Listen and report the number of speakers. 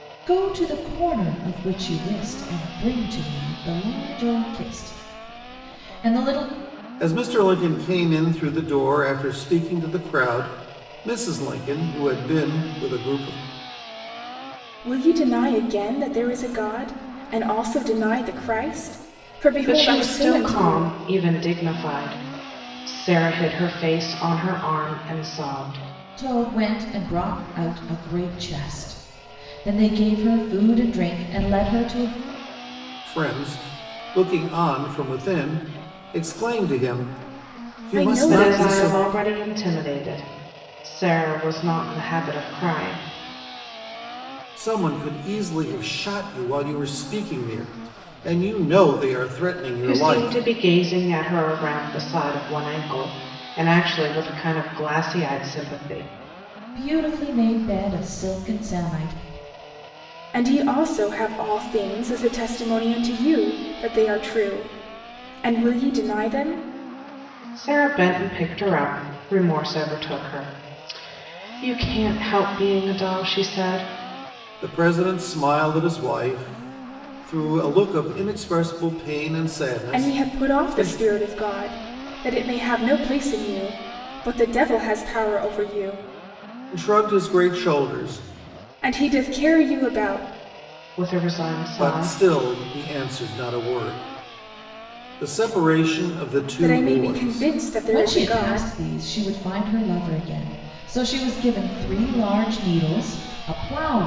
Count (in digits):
4